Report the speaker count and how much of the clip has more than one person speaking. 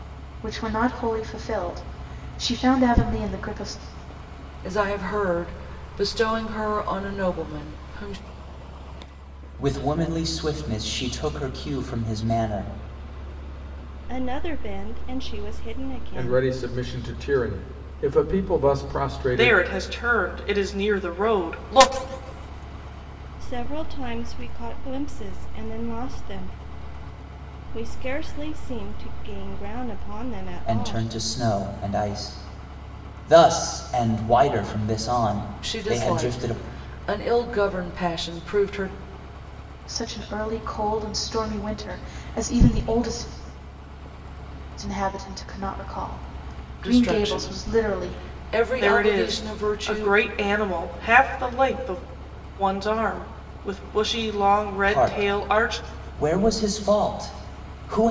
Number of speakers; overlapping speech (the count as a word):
six, about 10%